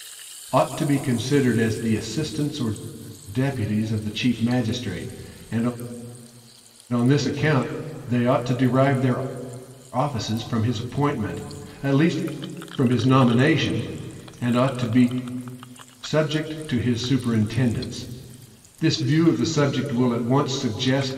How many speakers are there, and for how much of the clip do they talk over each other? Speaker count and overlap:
one, no overlap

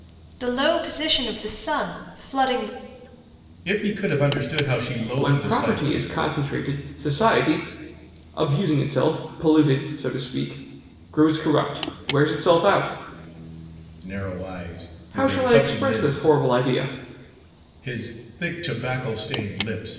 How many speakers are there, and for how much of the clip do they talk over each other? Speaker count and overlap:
three, about 11%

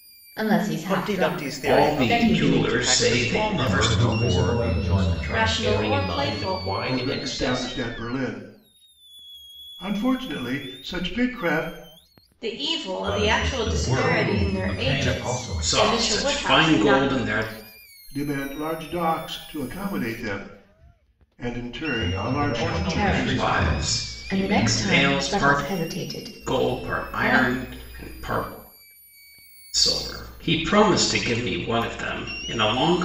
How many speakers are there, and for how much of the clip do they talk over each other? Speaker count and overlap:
eight, about 48%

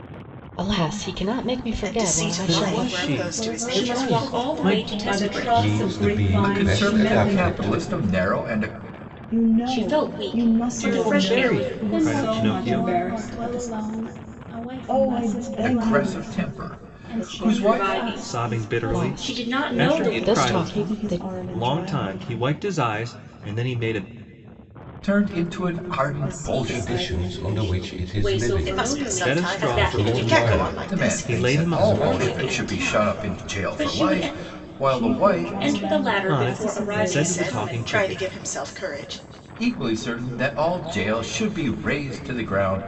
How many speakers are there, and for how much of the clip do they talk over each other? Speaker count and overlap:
nine, about 67%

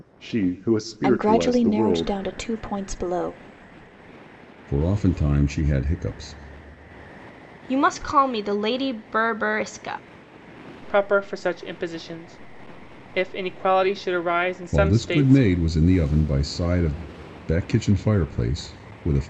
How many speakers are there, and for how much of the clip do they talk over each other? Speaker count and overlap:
five, about 10%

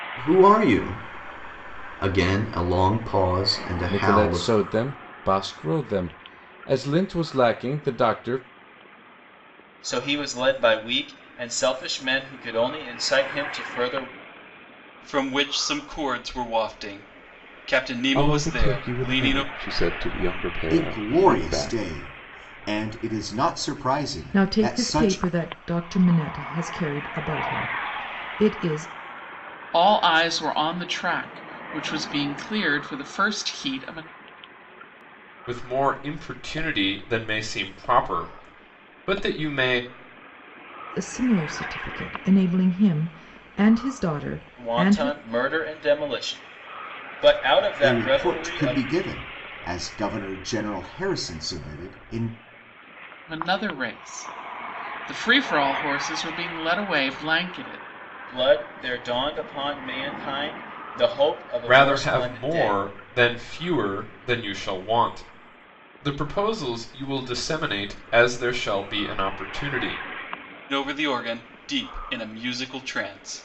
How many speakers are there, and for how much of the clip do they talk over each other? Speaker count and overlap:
nine, about 10%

